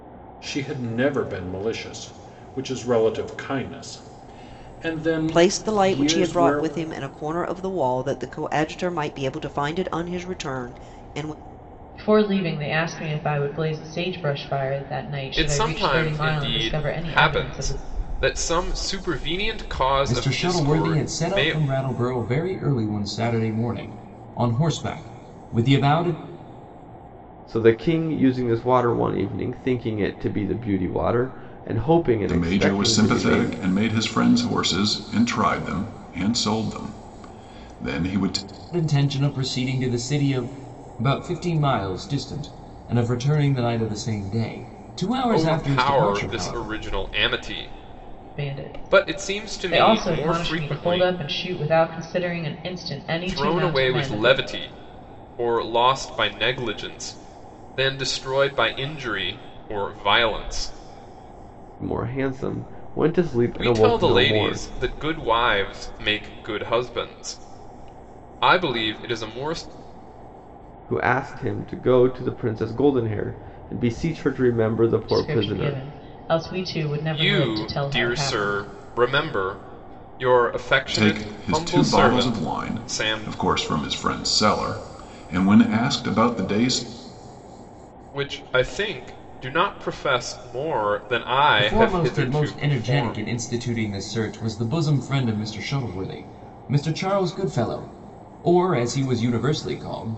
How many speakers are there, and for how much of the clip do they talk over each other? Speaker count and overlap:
7, about 20%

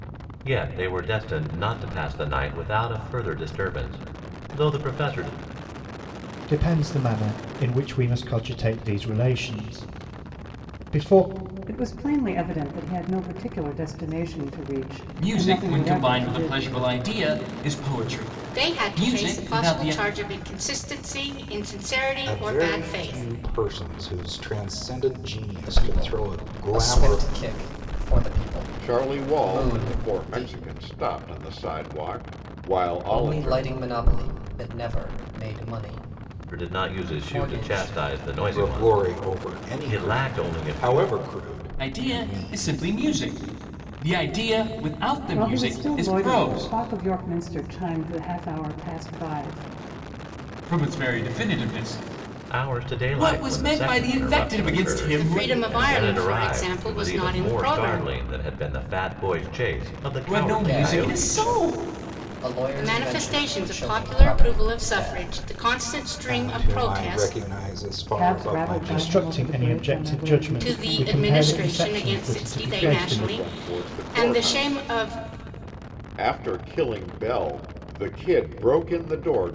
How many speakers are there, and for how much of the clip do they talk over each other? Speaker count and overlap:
8, about 41%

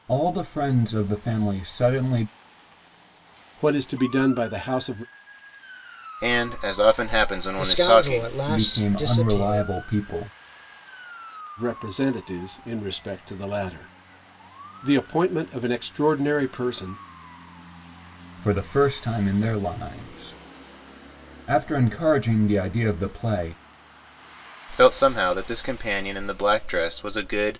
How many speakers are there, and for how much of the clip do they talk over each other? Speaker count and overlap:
4, about 8%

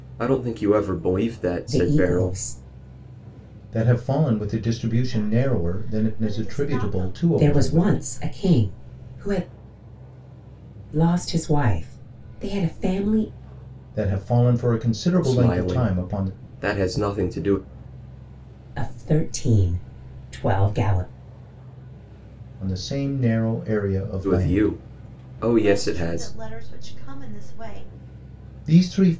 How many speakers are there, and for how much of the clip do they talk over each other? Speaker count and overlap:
4, about 21%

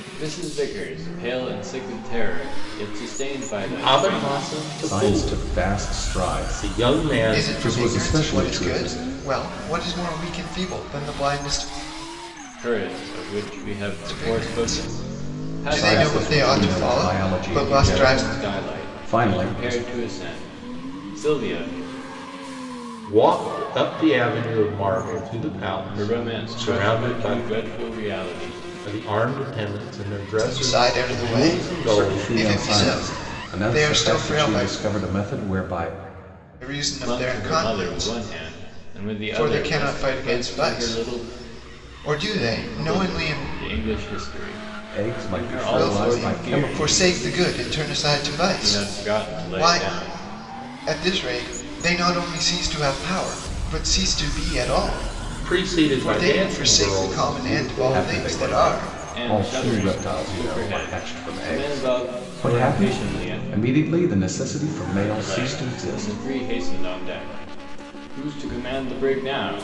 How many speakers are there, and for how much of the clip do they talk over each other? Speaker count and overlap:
4, about 47%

